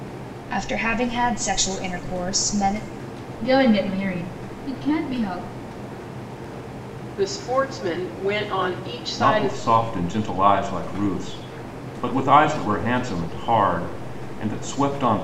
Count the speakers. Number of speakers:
four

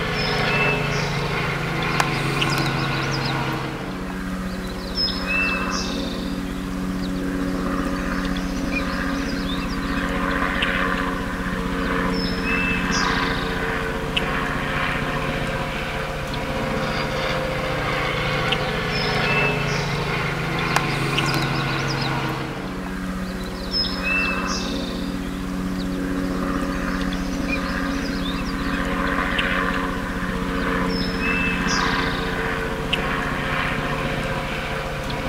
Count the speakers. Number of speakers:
zero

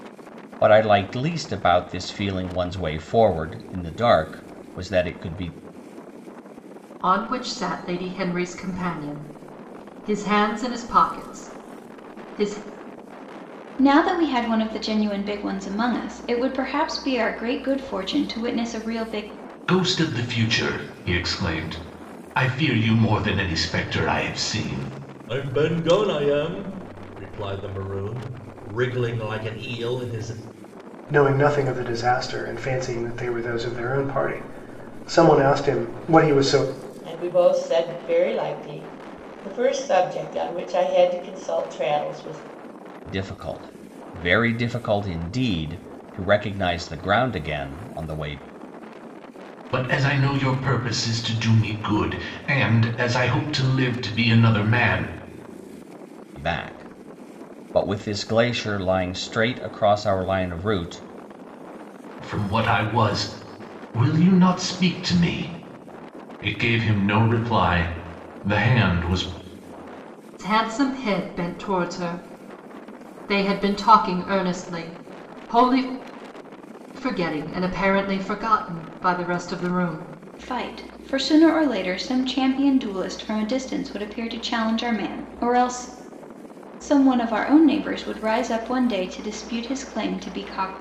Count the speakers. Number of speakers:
seven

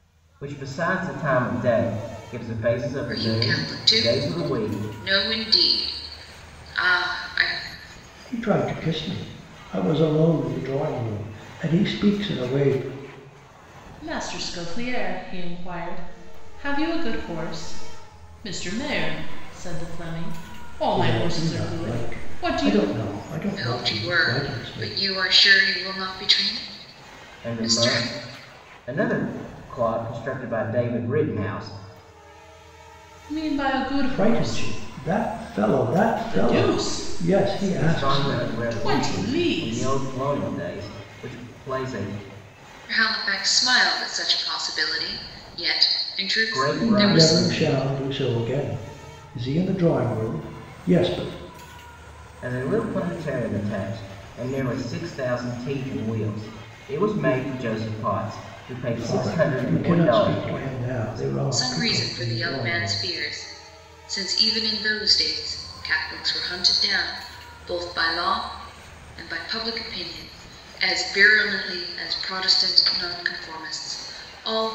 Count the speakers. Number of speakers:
four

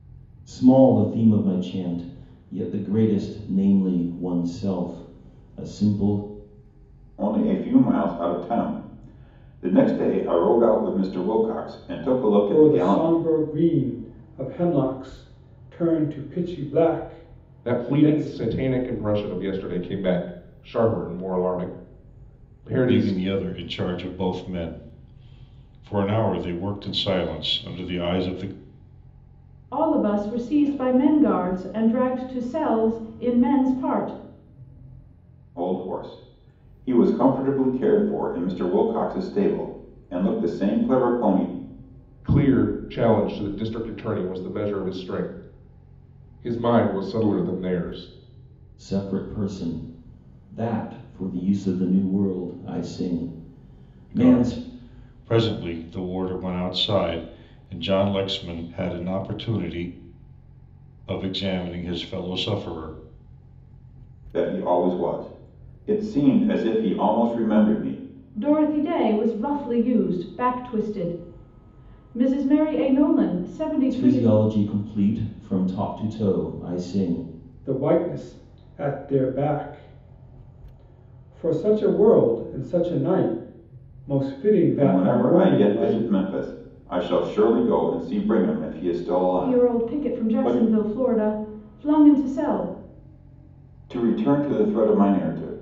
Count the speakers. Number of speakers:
six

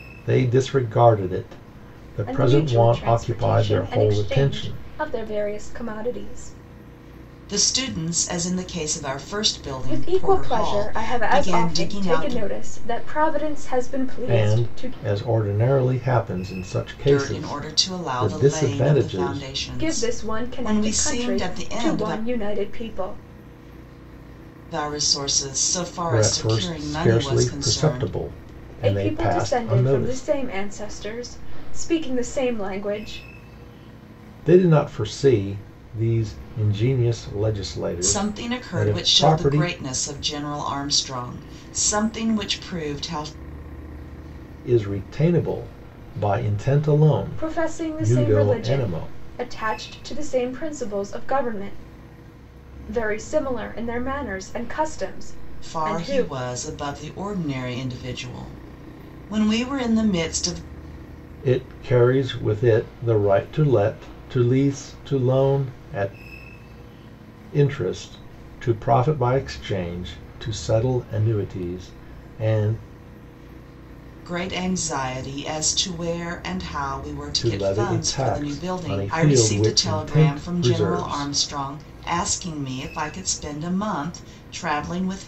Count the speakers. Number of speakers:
three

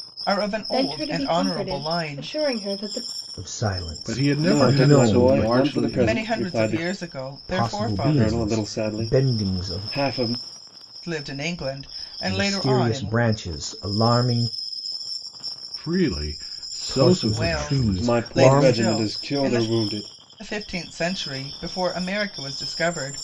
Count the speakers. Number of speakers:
five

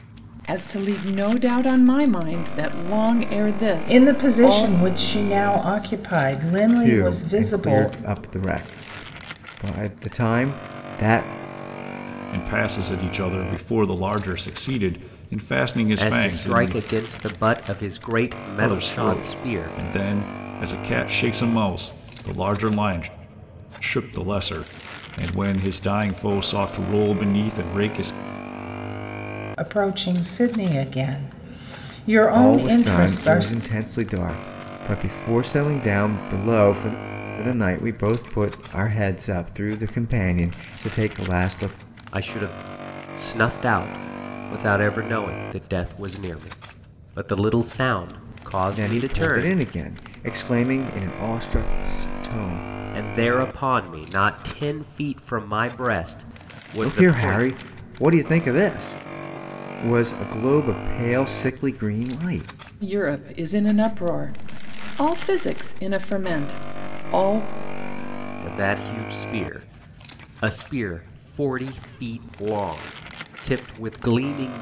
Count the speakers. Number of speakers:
five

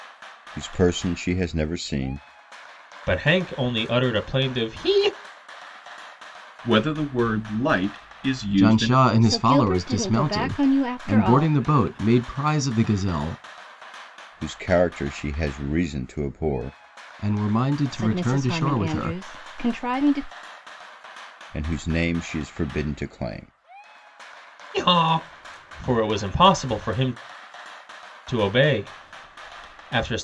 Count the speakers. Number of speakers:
five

